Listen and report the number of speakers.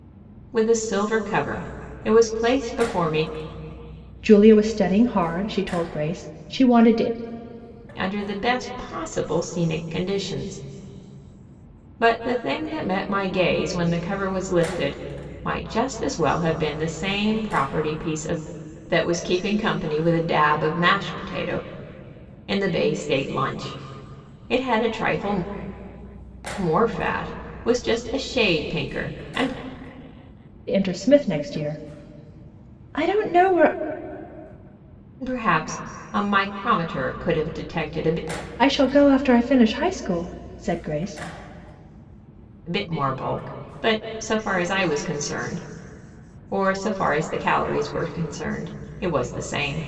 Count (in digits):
2